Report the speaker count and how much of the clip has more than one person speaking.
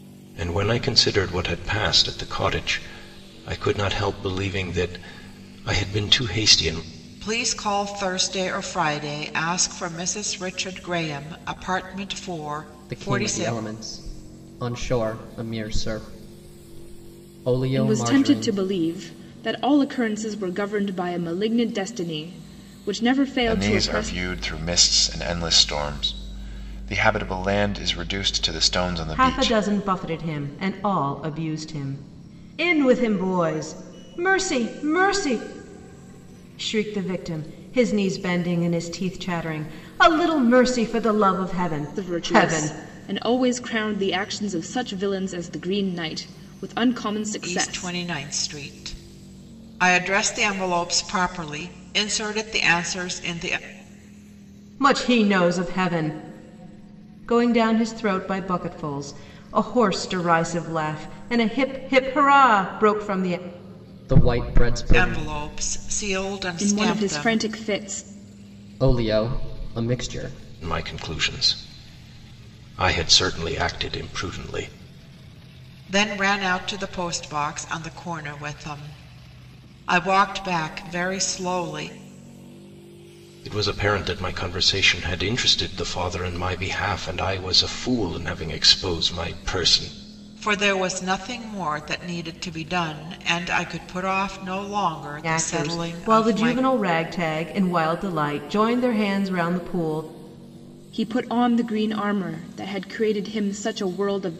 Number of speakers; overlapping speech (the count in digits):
6, about 7%